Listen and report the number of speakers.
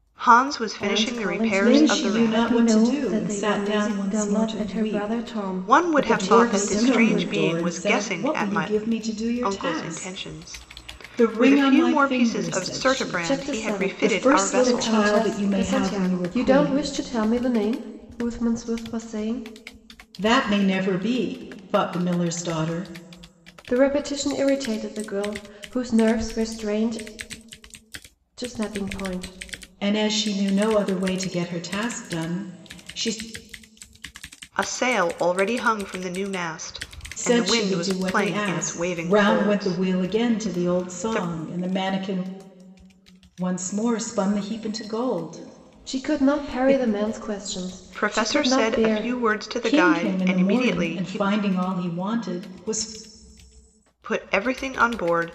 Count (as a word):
three